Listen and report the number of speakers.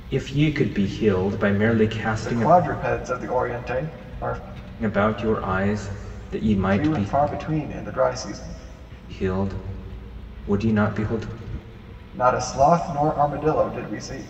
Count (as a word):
two